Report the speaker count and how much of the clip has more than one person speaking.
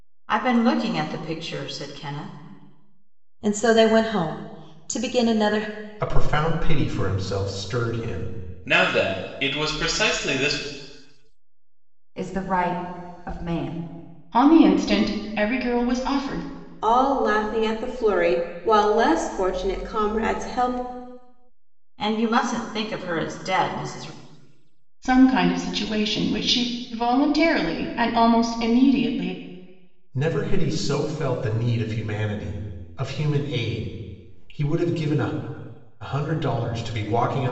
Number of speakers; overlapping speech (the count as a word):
seven, no overlap